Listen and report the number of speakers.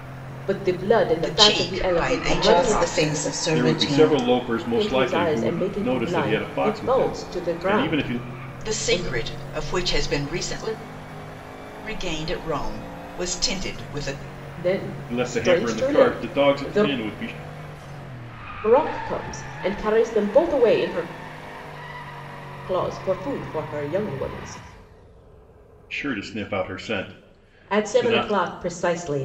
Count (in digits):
4